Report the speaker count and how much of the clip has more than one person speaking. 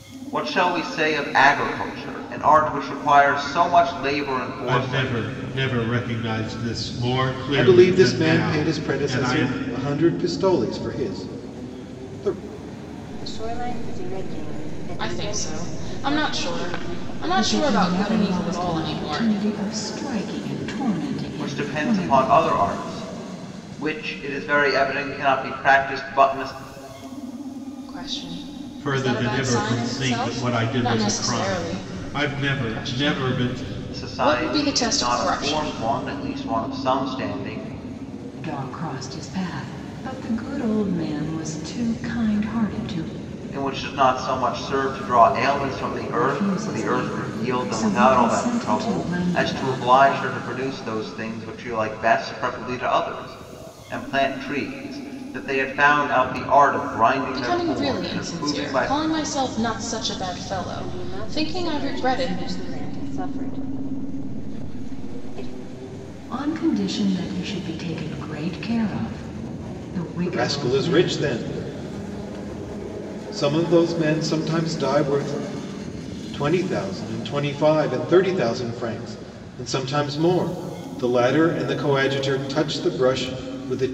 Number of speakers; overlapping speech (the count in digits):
6, about 27%